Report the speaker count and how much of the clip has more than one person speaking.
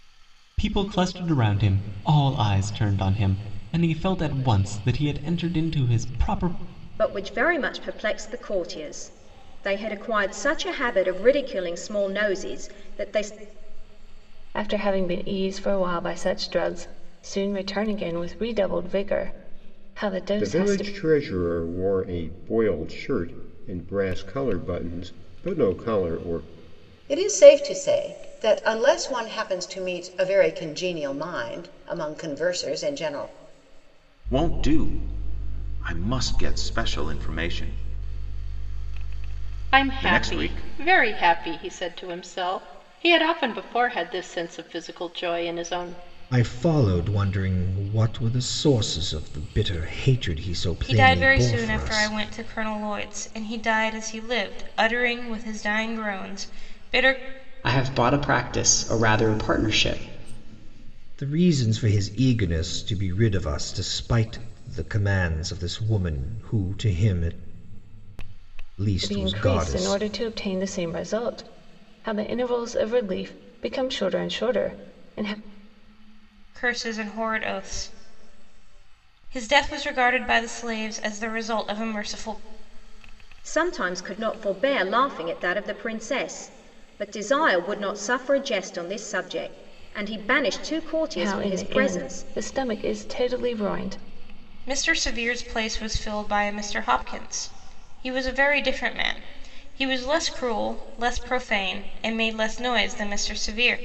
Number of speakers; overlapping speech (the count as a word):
ten, about 5%